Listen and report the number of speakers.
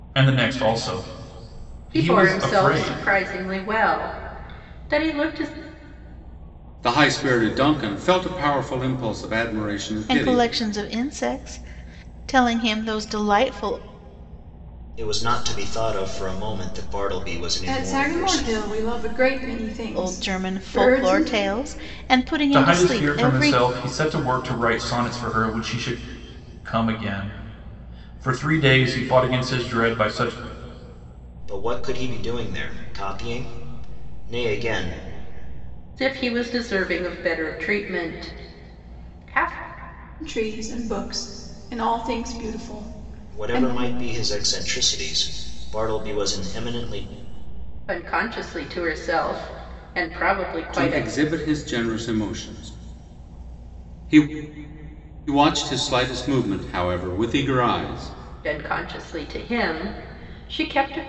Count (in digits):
6